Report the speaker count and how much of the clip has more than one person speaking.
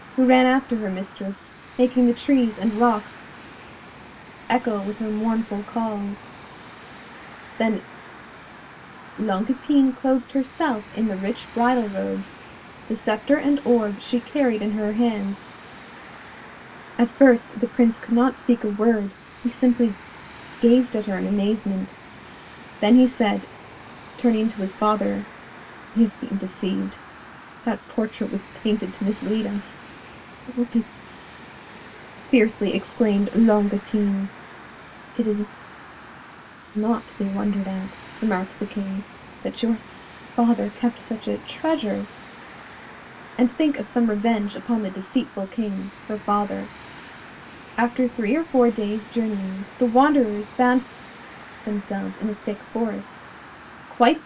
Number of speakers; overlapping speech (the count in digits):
1, no overlap